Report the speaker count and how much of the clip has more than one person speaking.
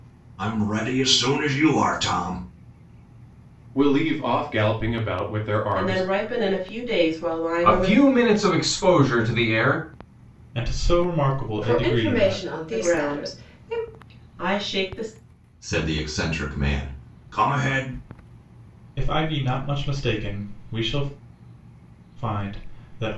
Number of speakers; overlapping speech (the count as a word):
six, about 12%